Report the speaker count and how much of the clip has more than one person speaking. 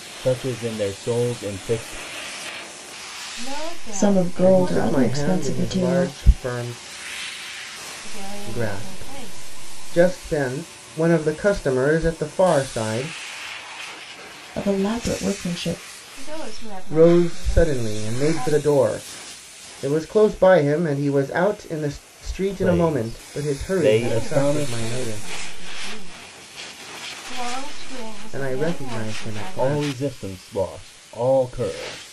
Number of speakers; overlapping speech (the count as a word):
four, about 33%